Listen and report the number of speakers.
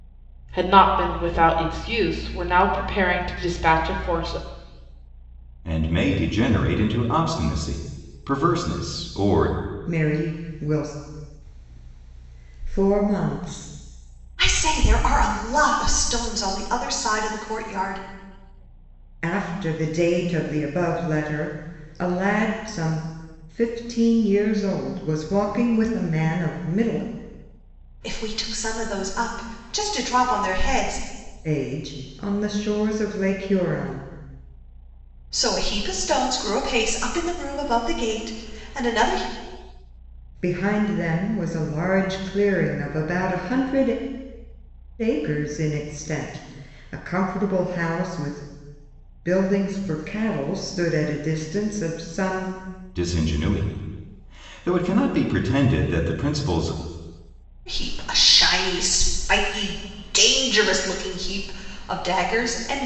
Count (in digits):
4